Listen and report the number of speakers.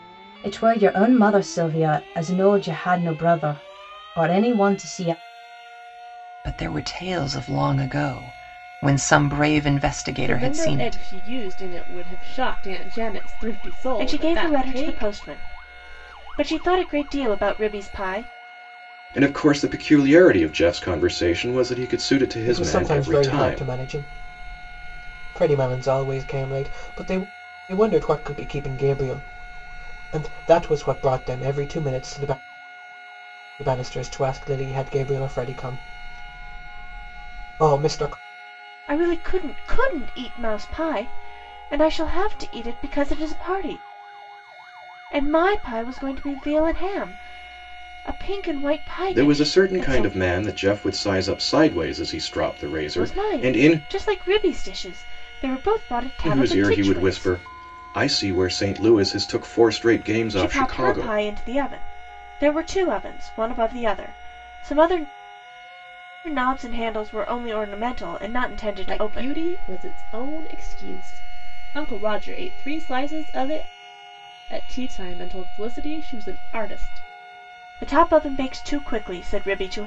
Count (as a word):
six